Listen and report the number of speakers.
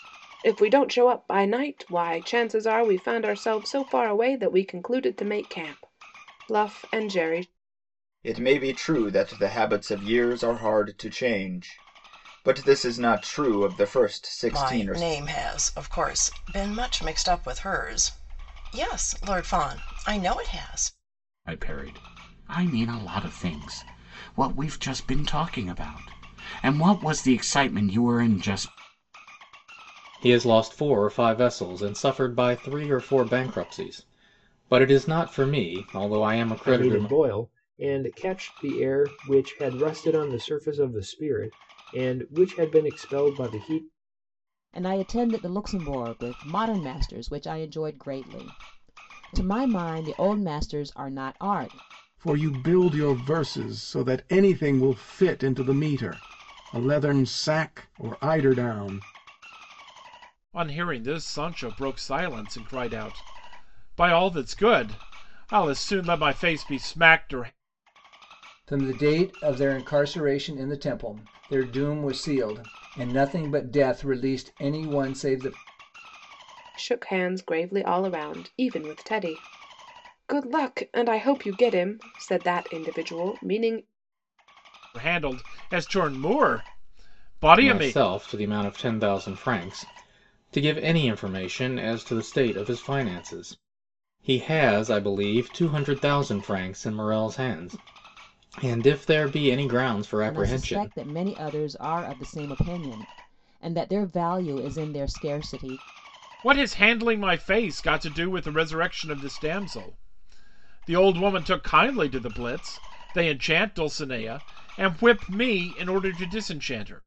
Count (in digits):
10